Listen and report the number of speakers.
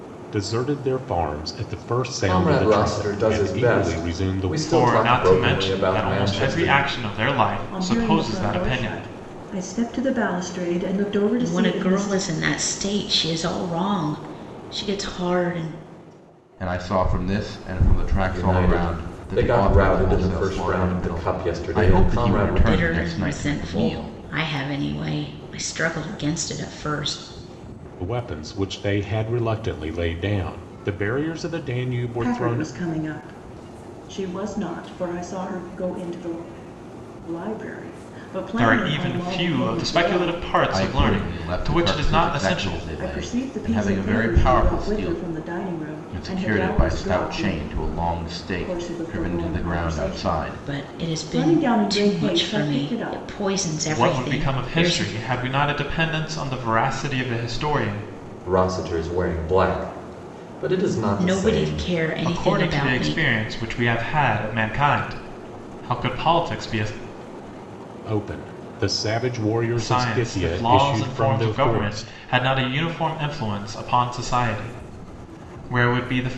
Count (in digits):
6